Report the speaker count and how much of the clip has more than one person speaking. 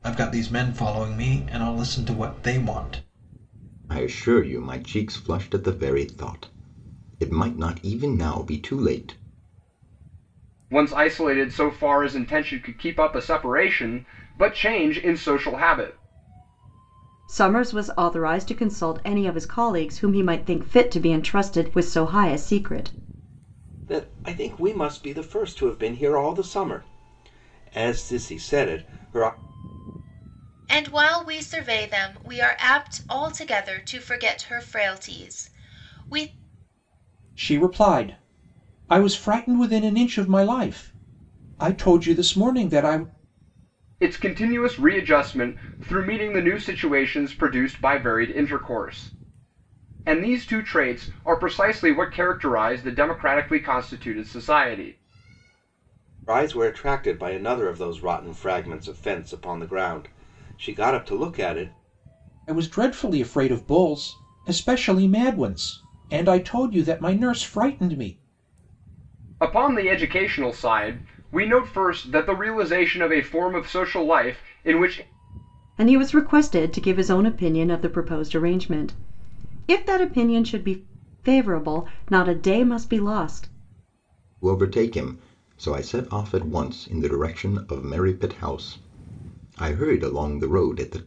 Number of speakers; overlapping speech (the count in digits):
7, no overlap